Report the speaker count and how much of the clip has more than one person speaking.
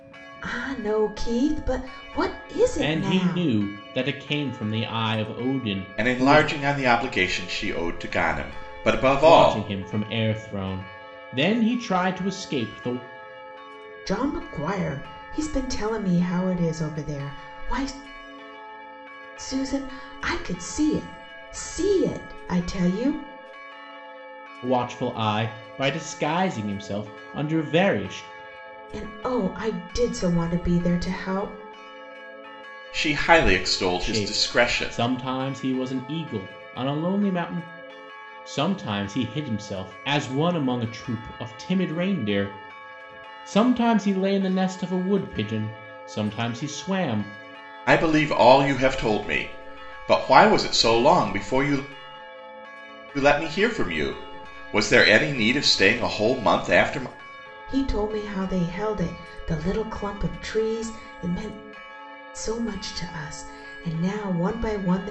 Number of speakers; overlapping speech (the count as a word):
three, about 4%